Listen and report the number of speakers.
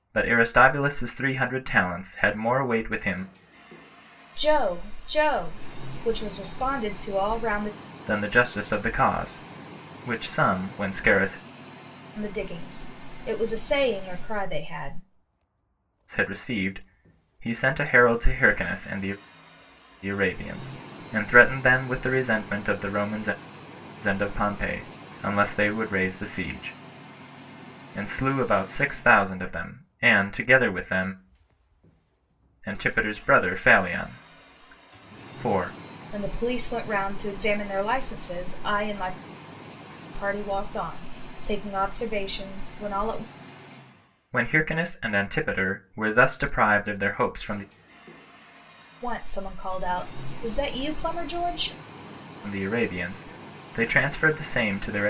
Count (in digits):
2